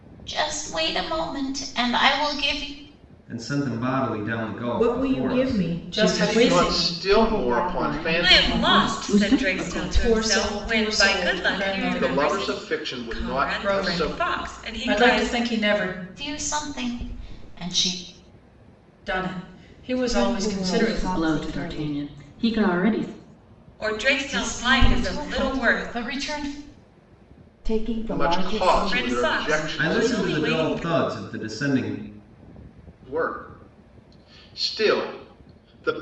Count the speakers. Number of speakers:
eight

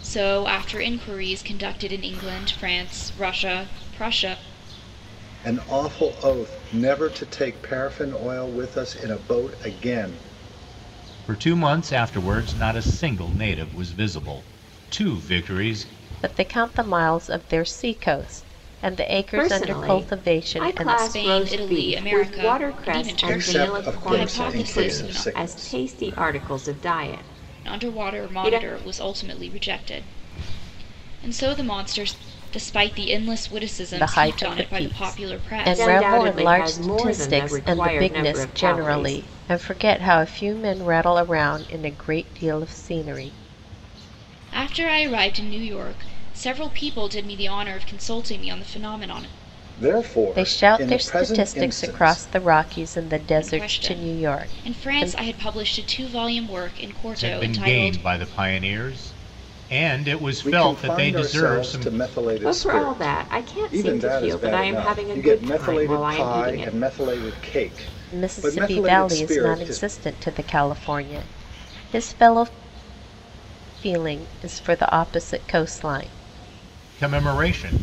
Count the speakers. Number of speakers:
five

